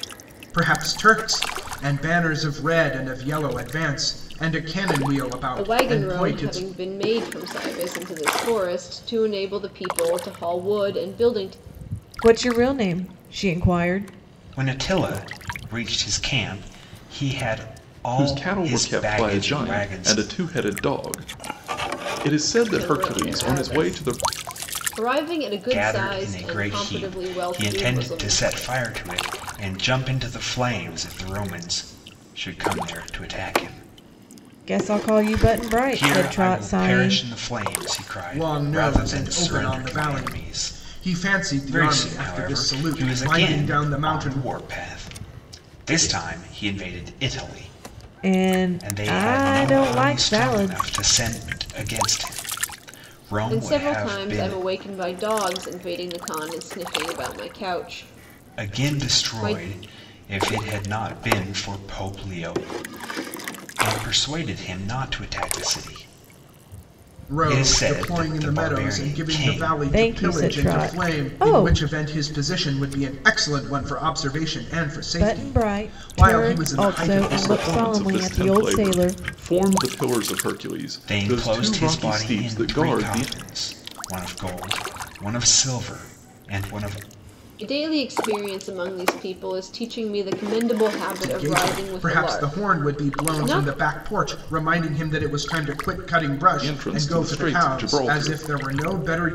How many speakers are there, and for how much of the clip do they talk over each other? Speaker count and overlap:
5, about 34%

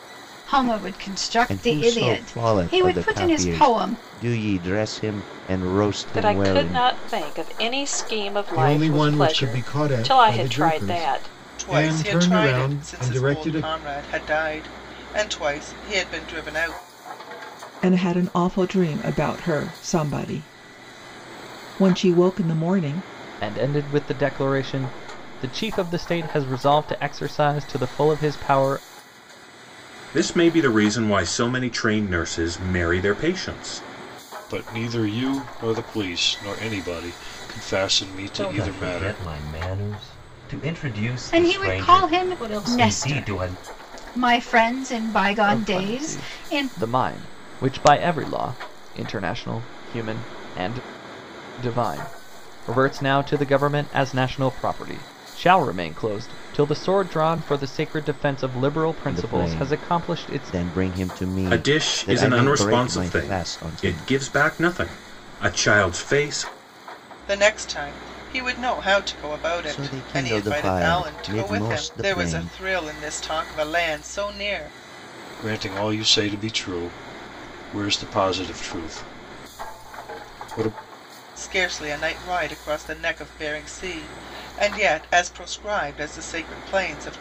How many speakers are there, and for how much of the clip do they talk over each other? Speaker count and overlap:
10, about 23%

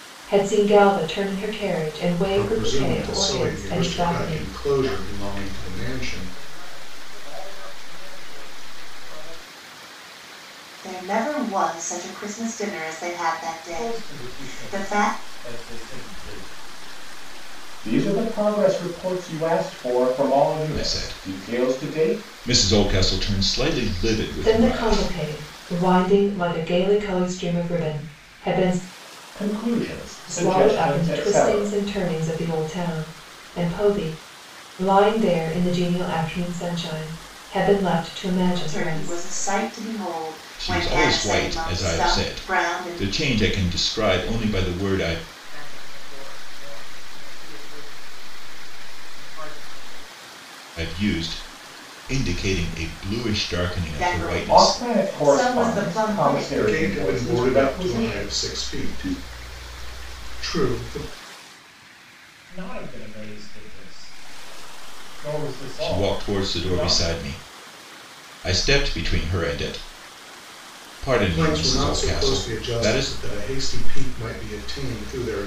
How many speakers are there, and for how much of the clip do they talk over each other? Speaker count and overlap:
7, about 29%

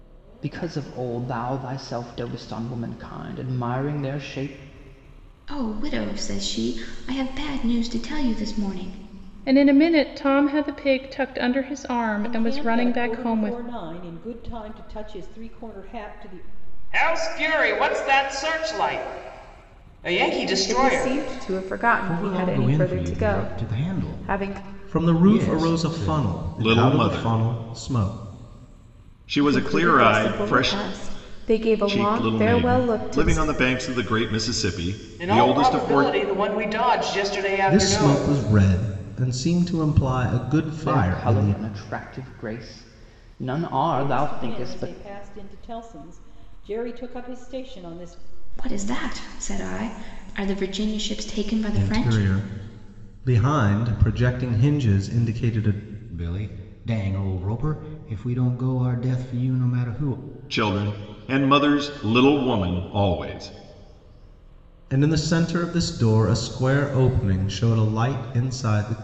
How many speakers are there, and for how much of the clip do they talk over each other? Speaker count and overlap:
9, about 22%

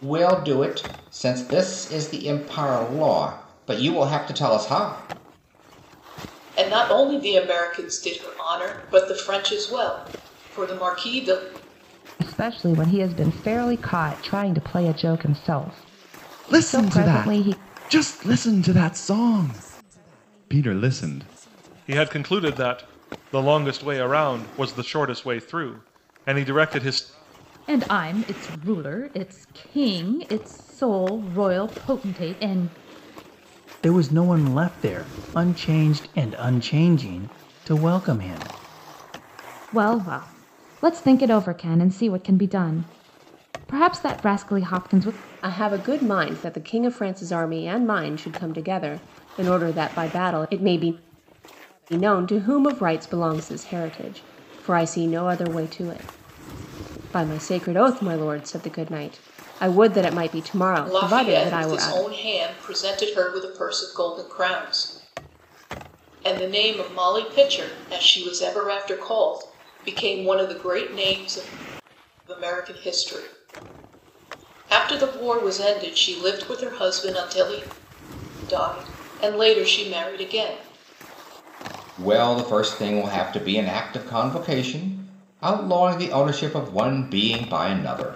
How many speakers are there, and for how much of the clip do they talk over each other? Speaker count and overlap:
9, about 3%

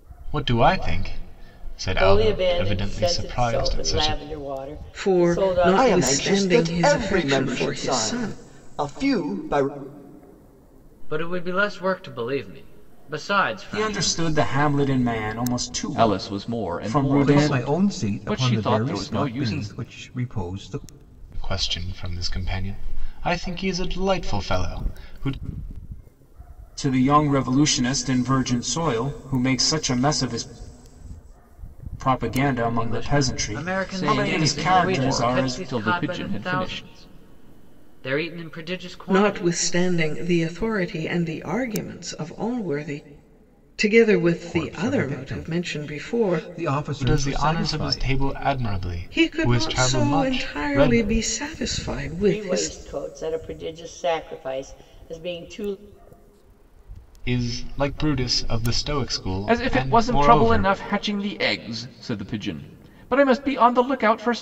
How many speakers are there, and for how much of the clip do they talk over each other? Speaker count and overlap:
8, about 34%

